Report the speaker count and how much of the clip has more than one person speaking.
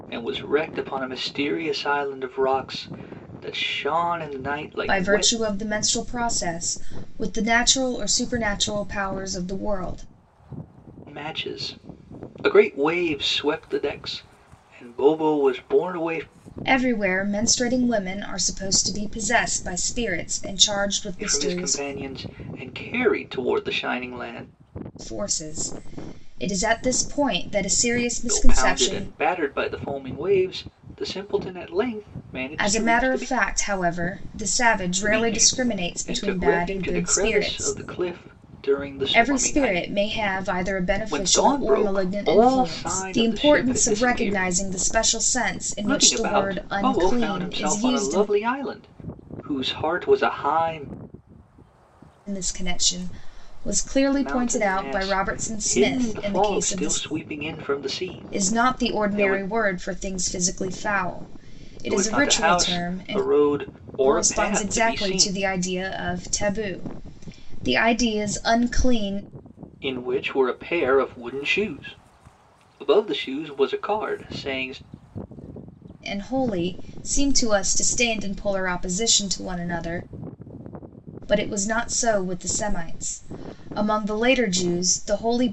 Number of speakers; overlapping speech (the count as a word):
two, about 23%